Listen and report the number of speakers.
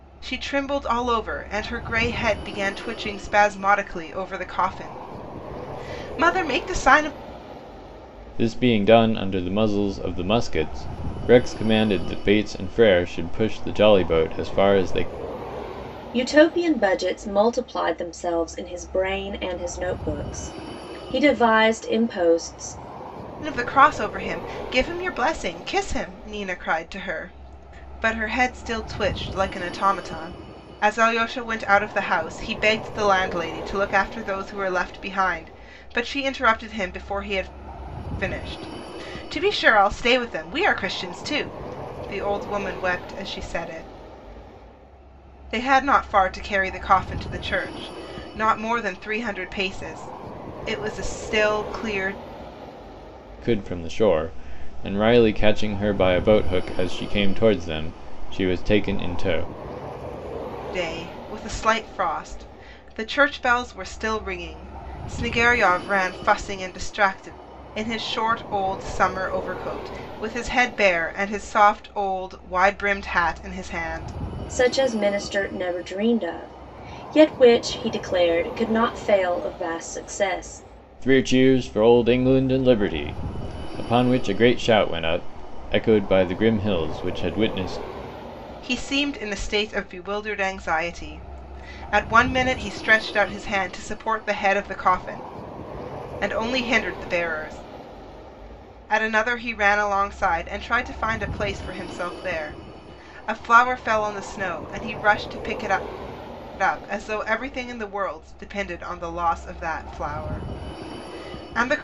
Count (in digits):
3